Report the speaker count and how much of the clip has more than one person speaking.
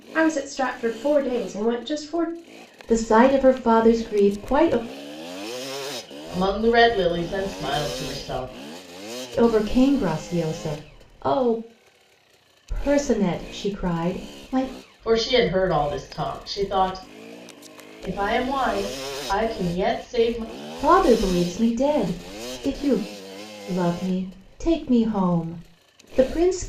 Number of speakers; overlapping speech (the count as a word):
three, no overlap